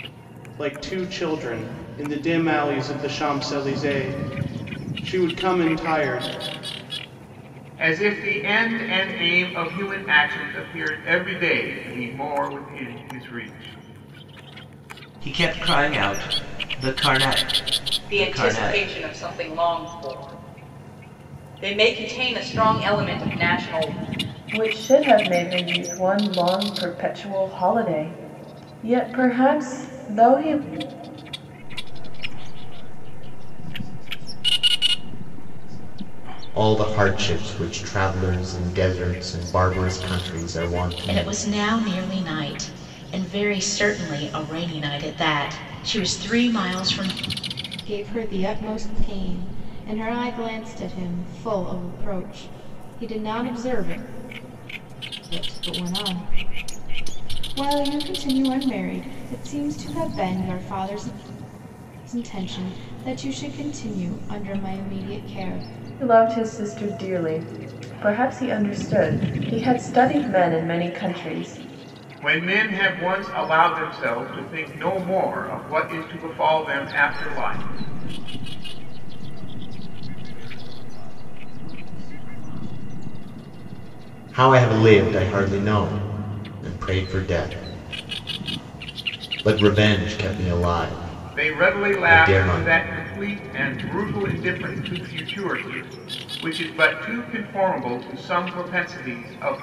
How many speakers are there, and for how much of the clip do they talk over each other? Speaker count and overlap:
nine, about 5%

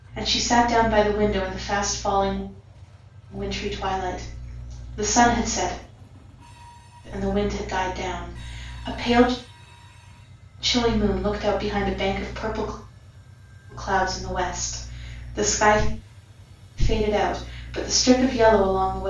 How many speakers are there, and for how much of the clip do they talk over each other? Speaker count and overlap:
one, no overlap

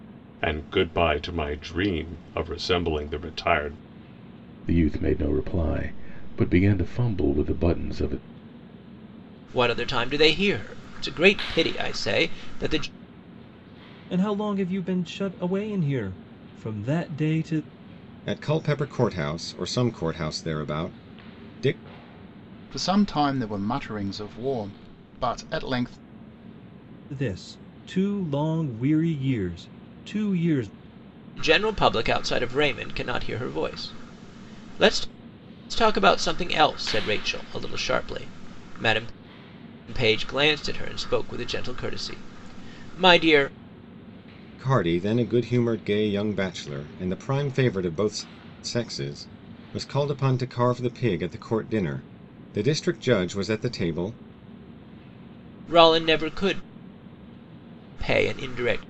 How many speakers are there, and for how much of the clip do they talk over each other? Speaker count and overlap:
six, no overlap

